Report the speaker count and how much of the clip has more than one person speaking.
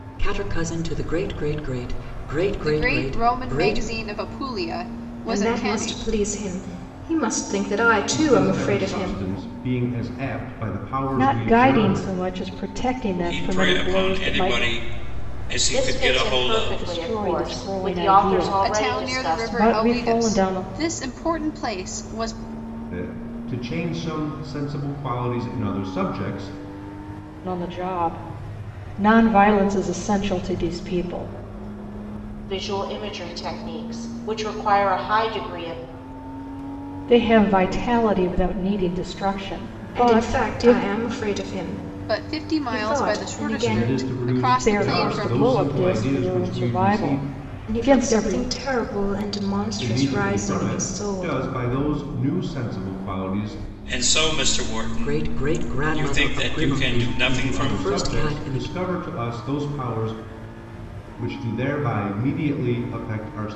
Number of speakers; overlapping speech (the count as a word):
seven, about 36%